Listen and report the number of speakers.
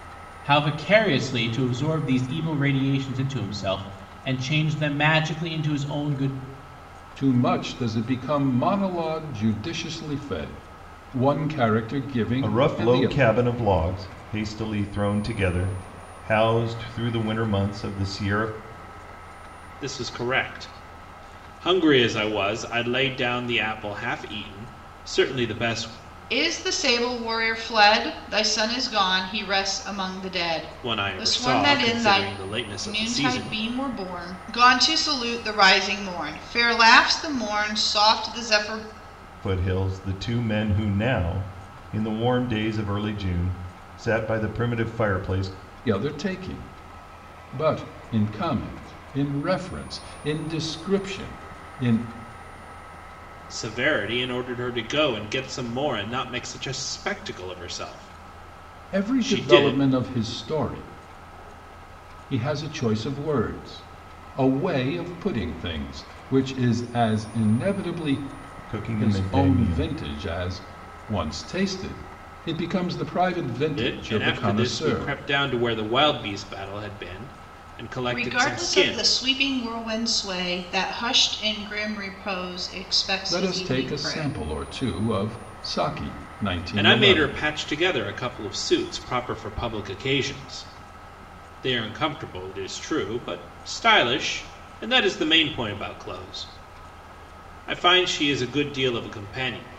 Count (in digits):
5